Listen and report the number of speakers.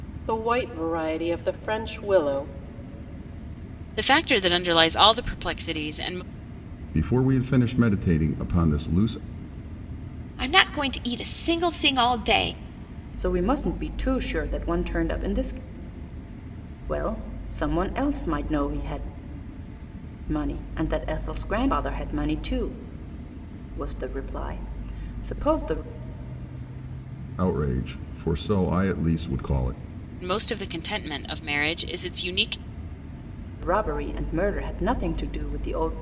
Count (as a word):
five